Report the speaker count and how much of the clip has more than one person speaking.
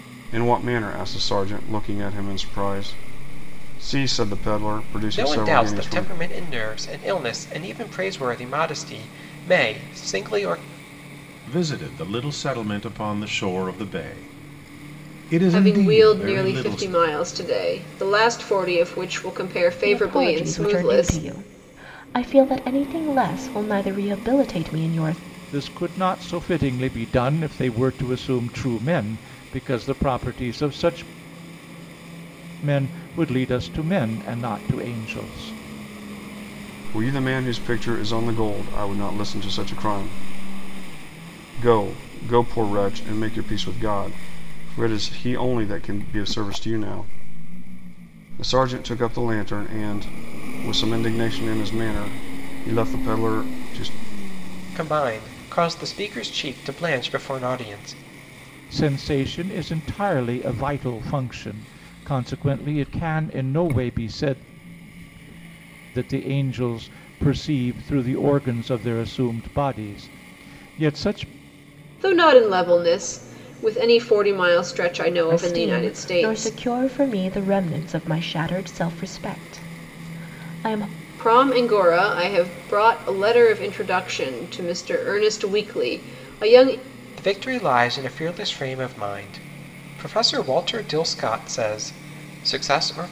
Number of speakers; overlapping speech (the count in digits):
6, about 5%